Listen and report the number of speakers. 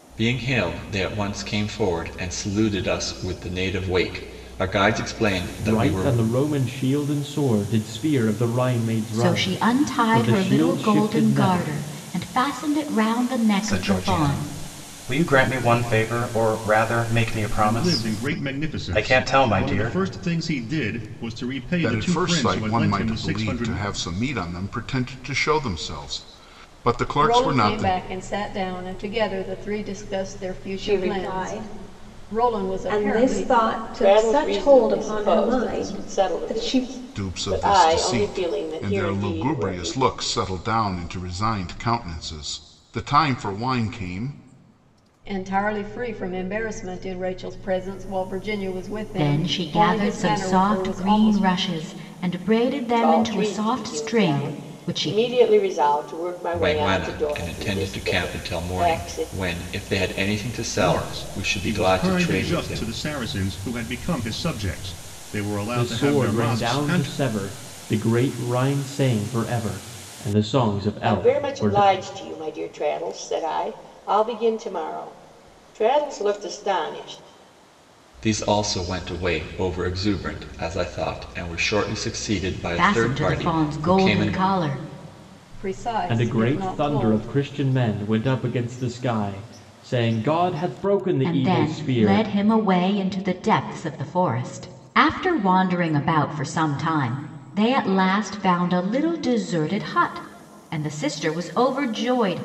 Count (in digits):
9